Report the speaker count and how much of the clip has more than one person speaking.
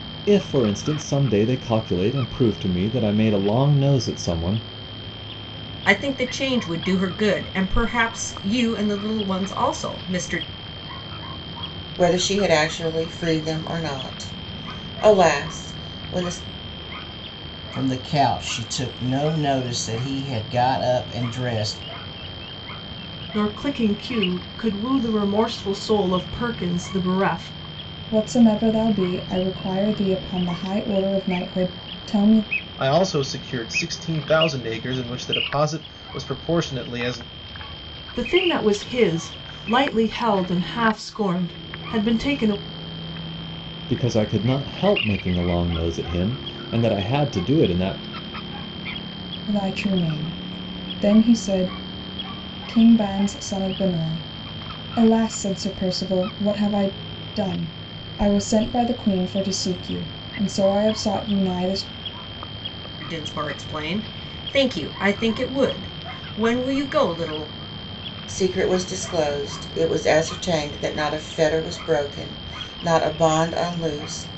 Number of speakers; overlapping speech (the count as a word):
seven, no overlap